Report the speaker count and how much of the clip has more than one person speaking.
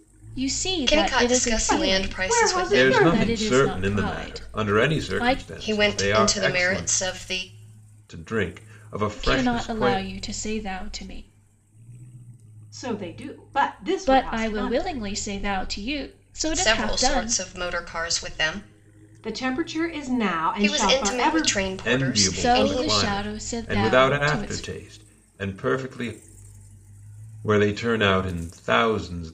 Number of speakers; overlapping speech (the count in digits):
4, about 44%